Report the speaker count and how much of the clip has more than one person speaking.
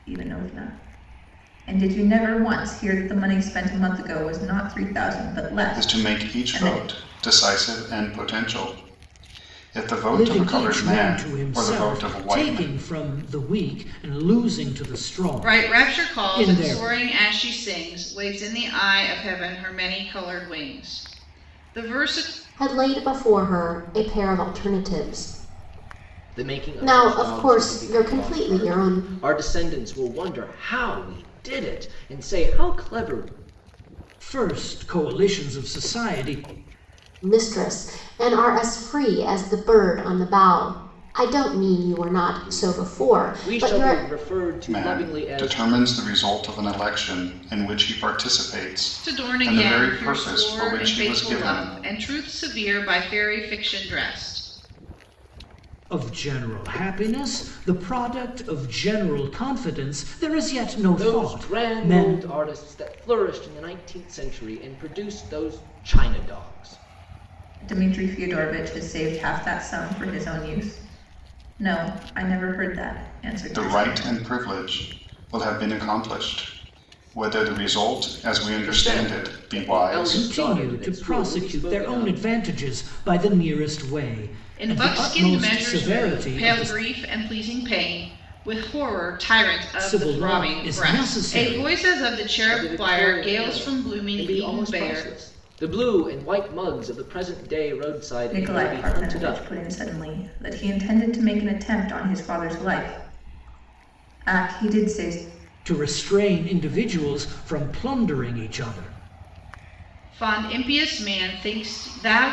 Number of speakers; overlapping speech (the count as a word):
six, about 24%